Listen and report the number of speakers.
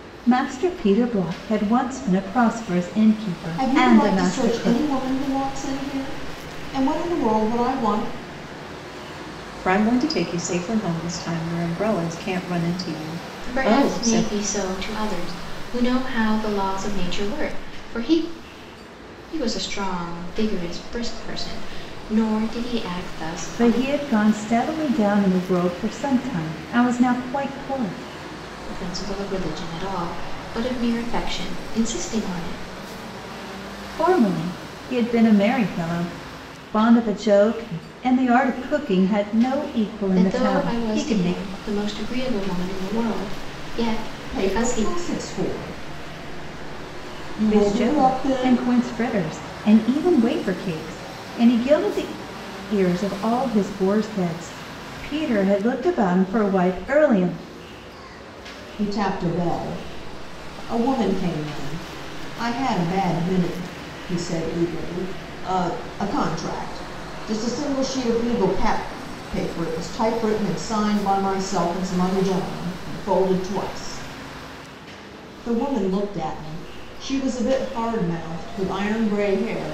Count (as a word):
four